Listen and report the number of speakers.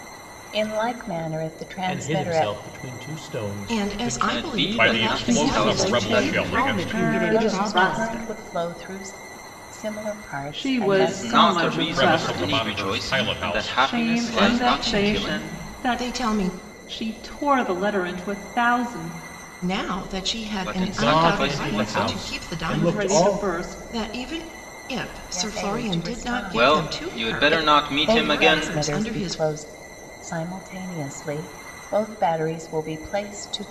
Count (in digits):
8